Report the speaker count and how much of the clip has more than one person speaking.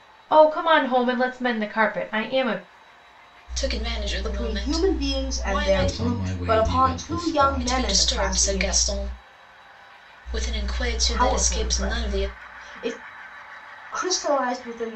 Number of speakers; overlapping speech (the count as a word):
four, about 40%